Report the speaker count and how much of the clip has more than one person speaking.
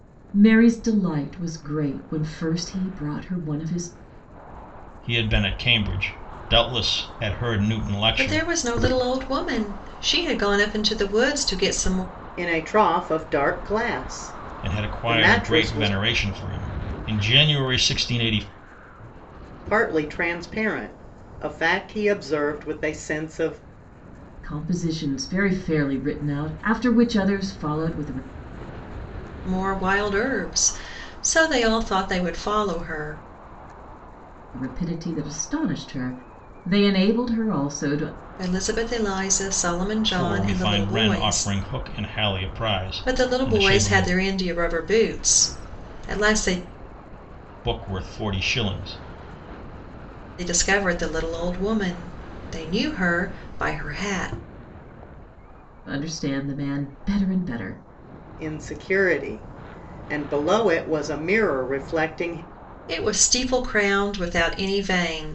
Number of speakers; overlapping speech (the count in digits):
4, about 7%